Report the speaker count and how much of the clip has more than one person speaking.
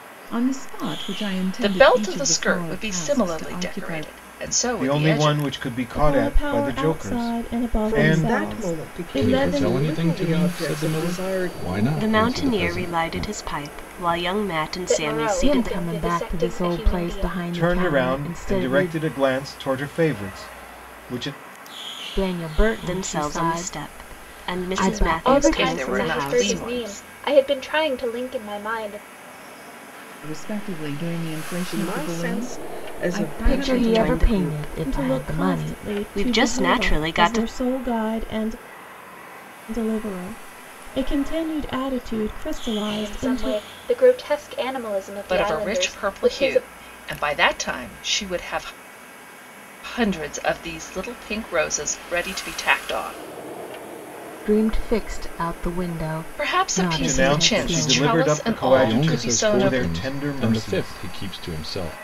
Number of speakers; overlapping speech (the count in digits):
9, about 50%